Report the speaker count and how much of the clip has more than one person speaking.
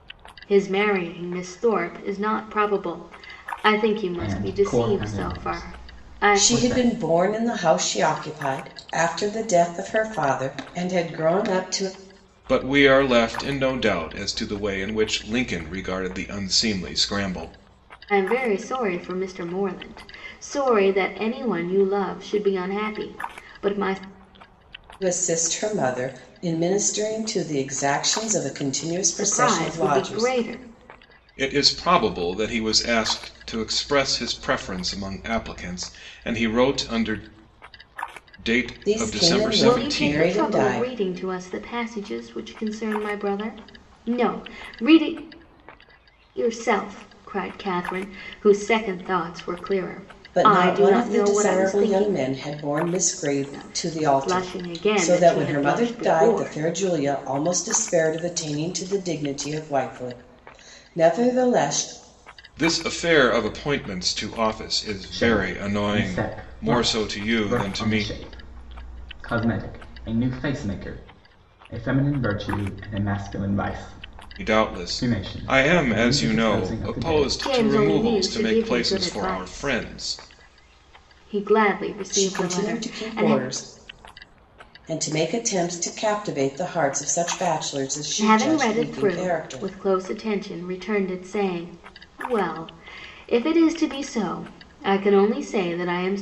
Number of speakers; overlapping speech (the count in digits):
4, about 24%